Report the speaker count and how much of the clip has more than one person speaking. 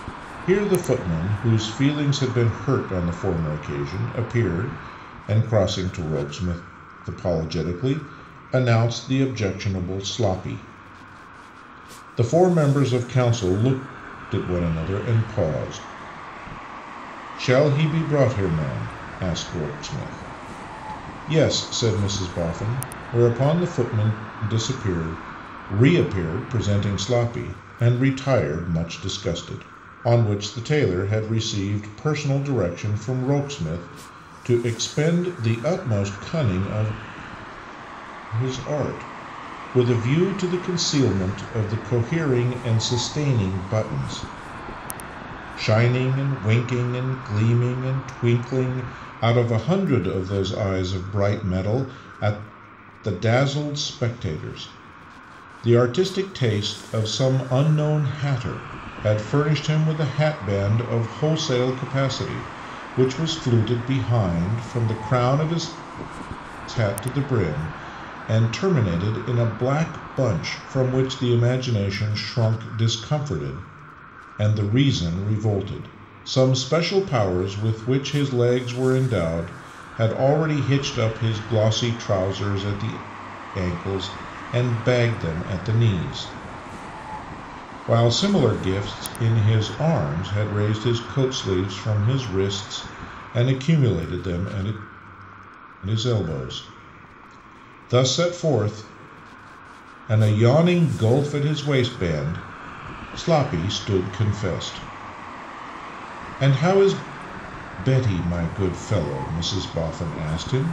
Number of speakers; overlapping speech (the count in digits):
1, no overlap